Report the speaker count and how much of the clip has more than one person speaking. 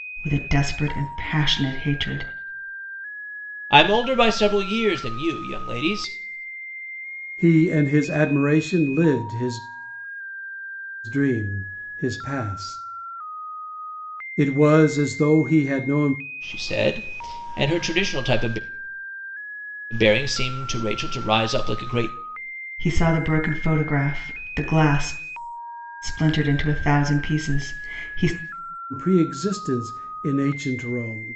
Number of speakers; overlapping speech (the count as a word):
three, no overlap